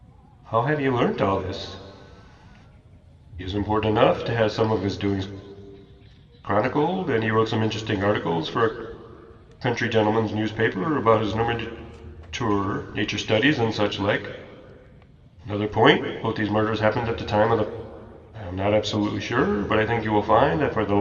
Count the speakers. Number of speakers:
1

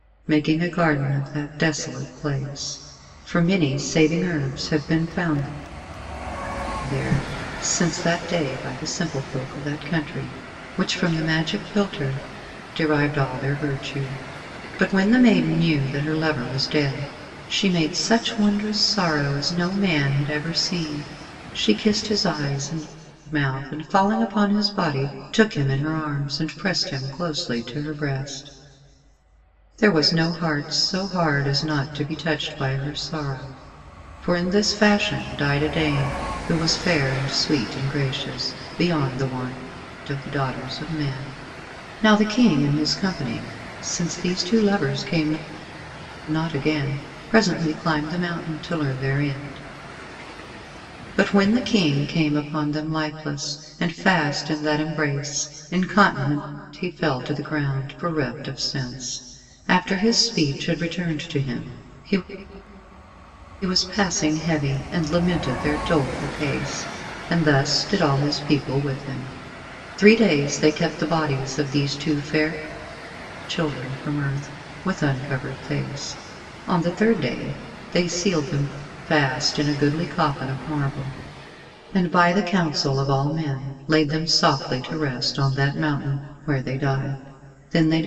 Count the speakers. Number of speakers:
1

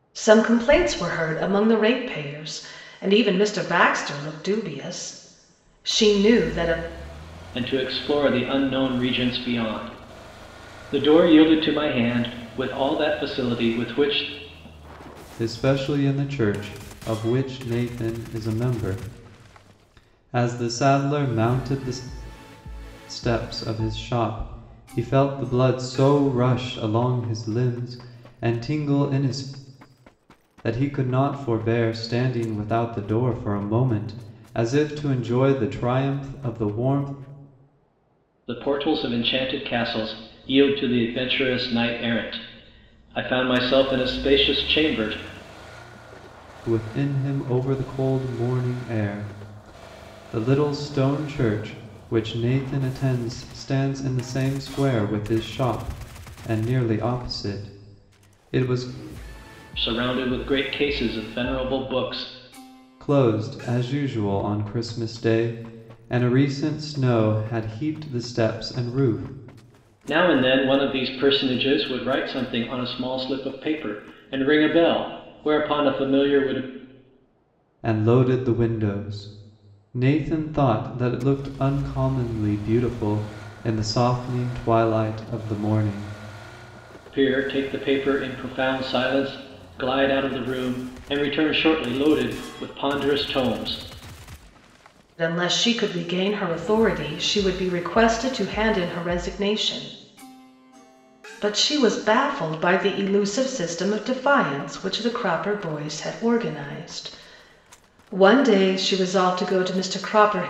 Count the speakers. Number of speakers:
3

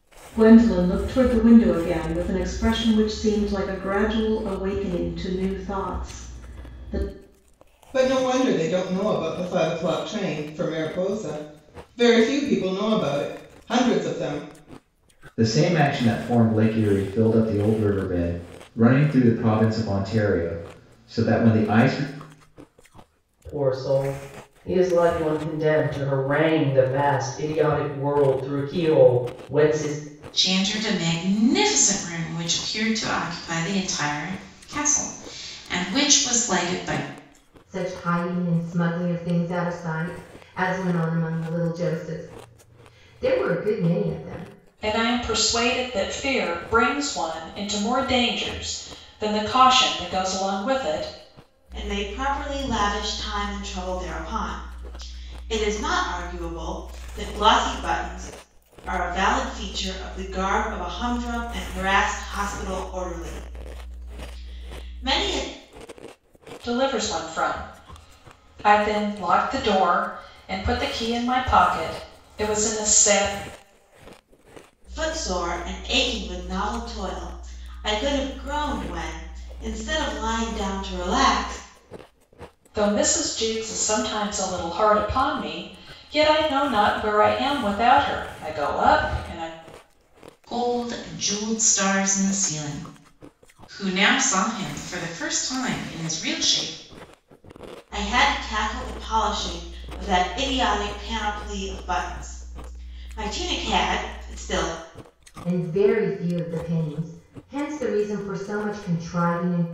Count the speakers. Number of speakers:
8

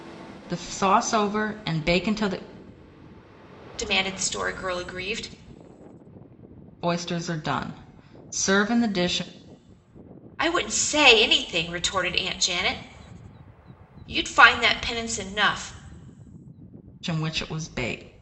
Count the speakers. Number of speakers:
2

